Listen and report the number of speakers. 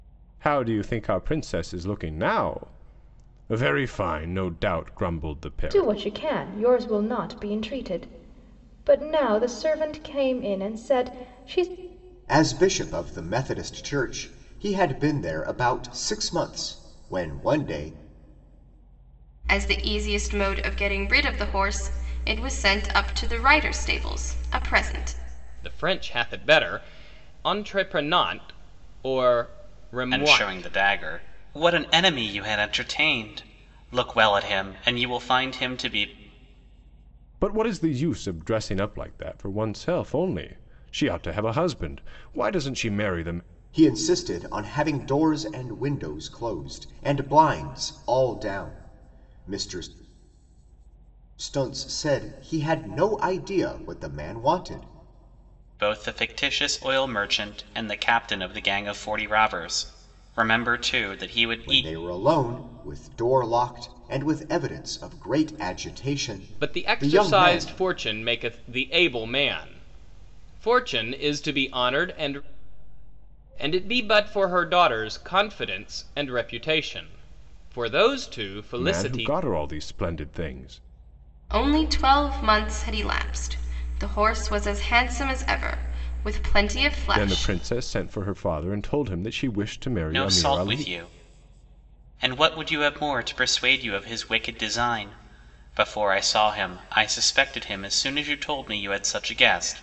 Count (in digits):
6